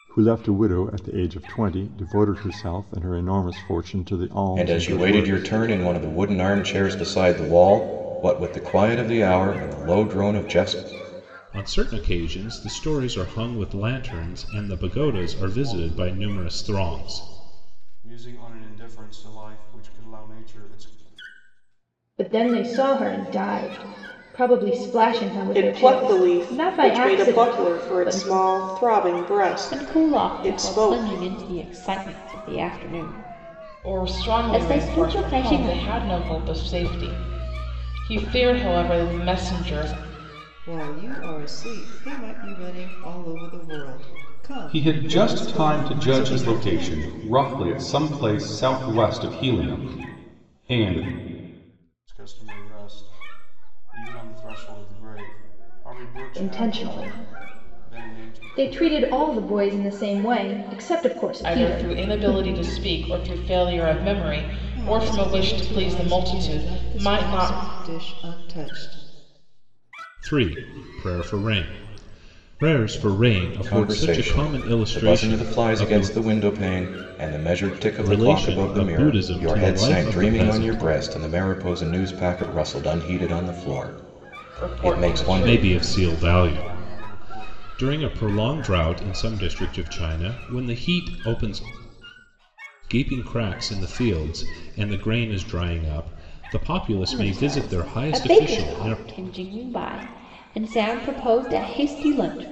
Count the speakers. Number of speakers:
ten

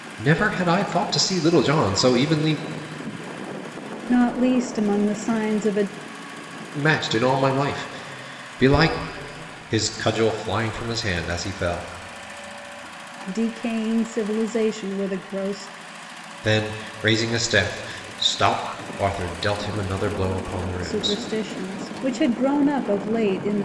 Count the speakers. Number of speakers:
two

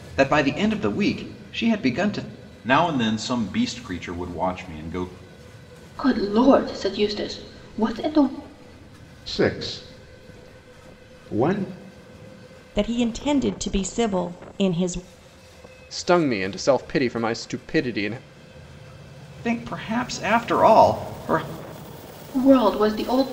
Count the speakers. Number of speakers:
six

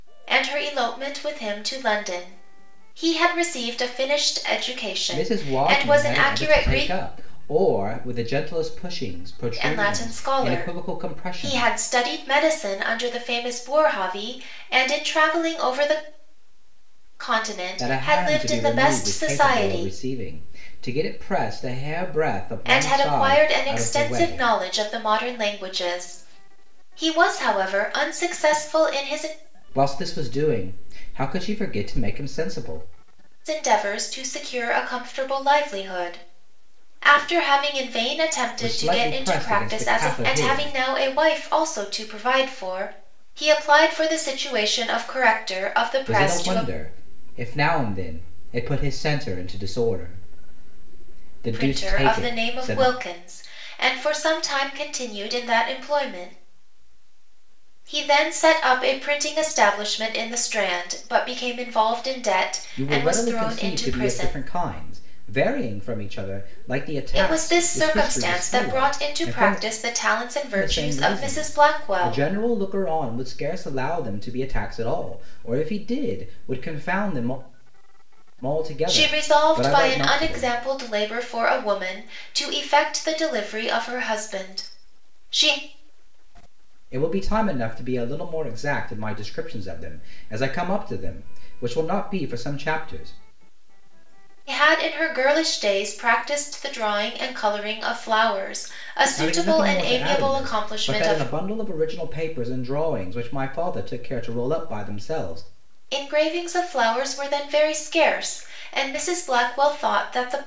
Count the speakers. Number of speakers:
two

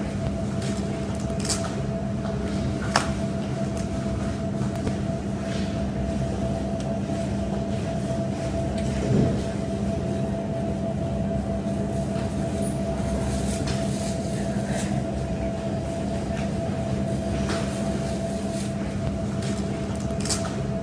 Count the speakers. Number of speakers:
zero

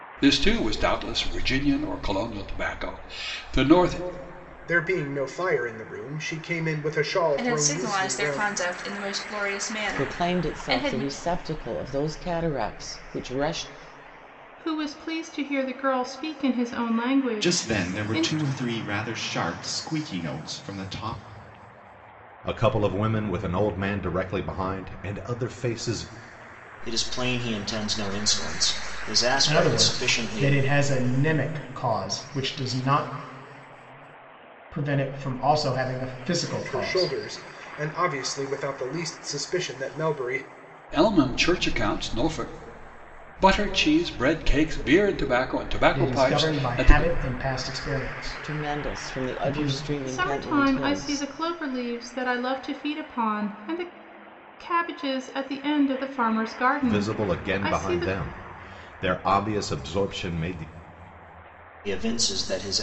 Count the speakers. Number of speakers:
nine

